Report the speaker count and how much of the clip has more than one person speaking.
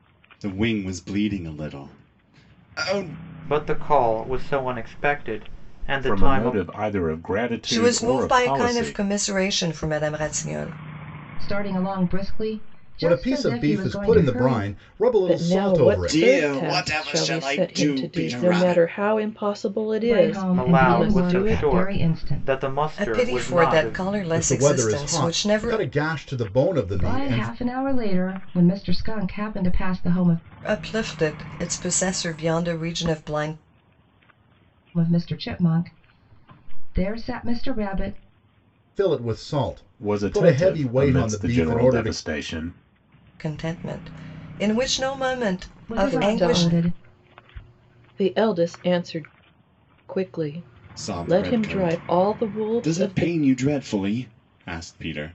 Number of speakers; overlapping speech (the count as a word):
seven, about 34%